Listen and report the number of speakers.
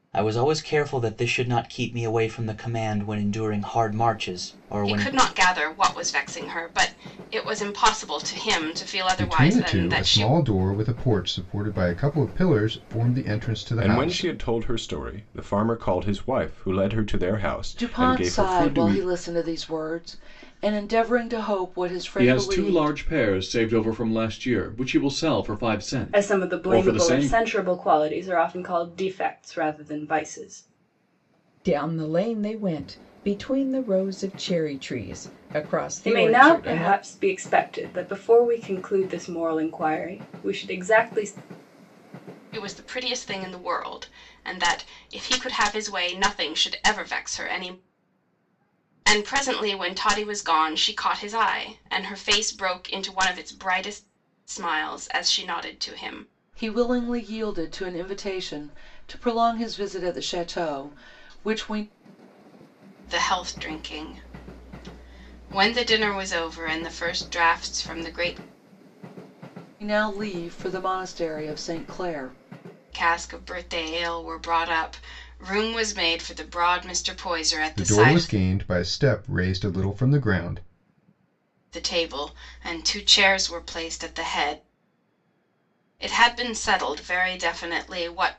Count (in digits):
8